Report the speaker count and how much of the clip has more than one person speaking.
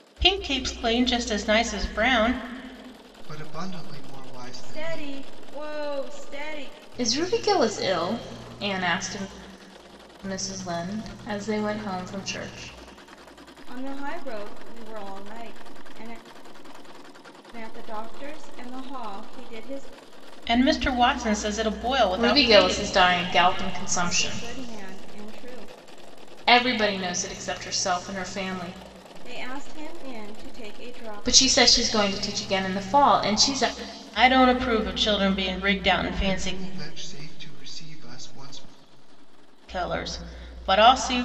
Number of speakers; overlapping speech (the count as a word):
four, about 8%